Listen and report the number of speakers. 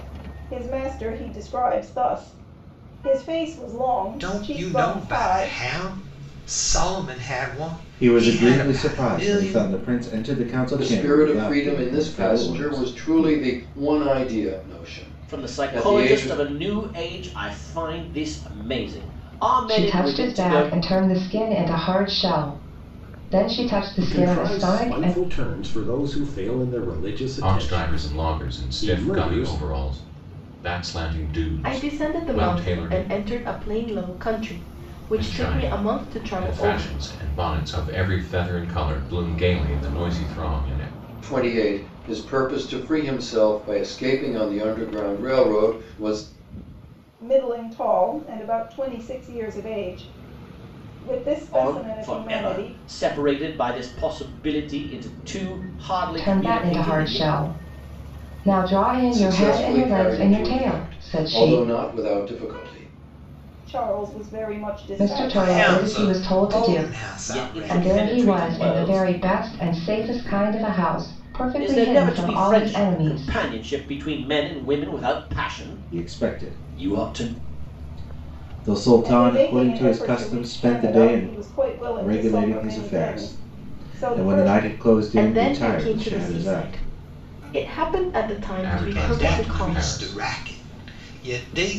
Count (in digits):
9